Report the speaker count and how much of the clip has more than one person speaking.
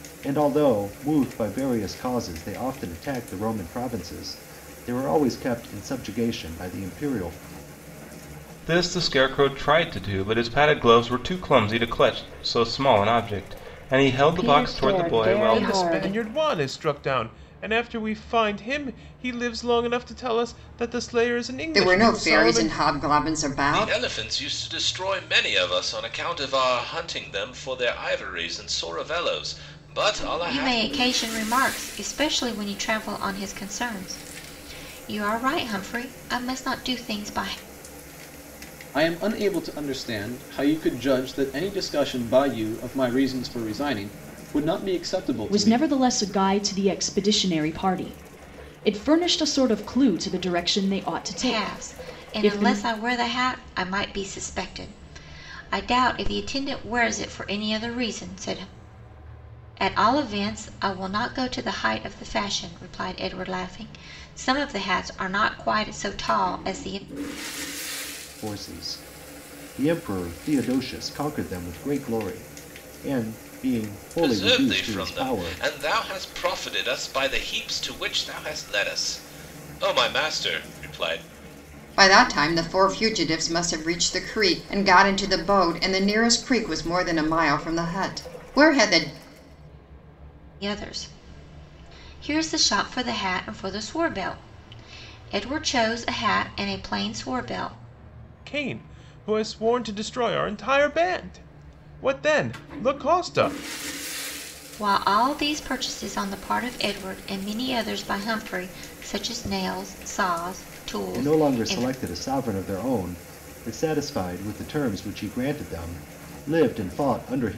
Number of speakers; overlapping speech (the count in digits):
9, about 7%